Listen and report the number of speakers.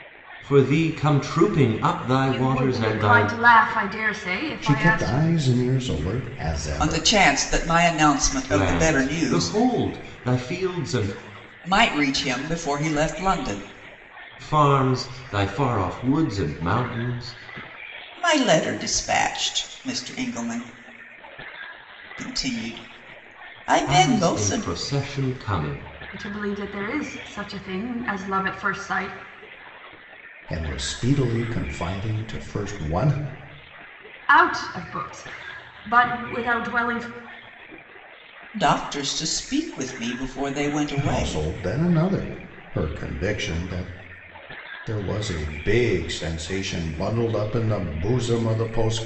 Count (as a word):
four